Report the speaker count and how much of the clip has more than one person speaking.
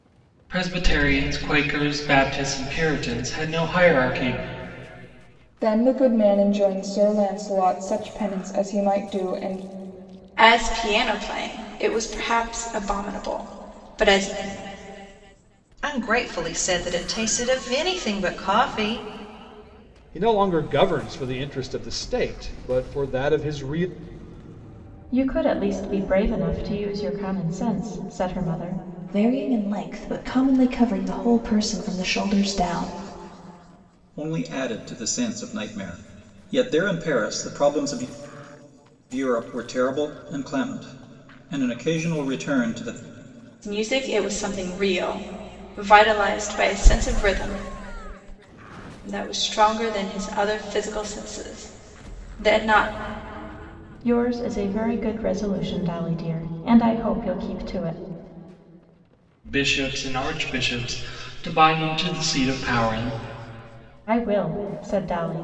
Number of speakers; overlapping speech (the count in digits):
8, no overlap